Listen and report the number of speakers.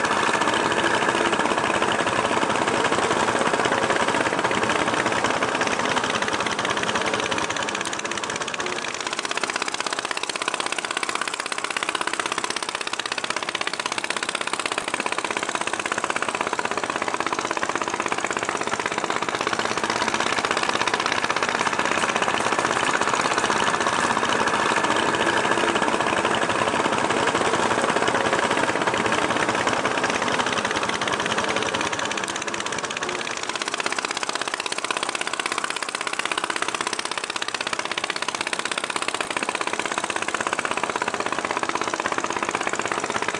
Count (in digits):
0